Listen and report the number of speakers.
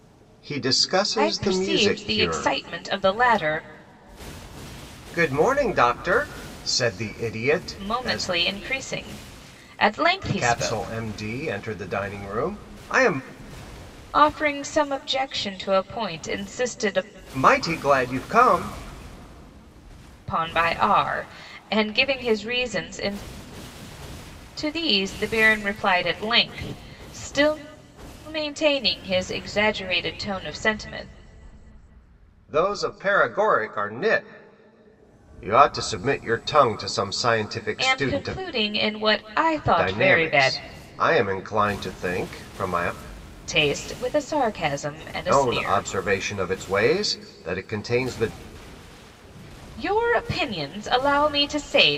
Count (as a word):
two